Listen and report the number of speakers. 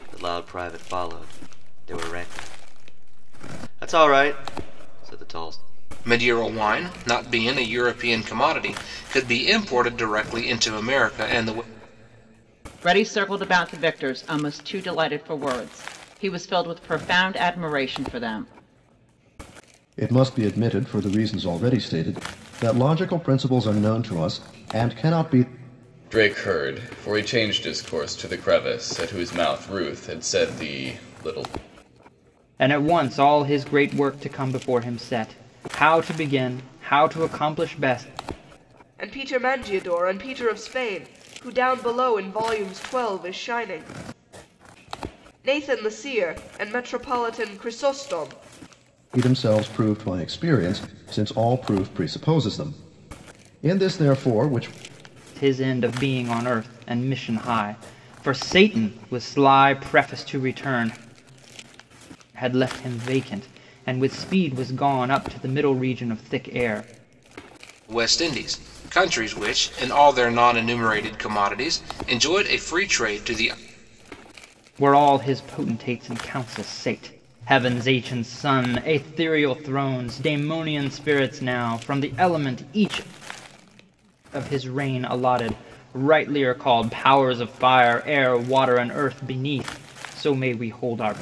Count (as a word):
seven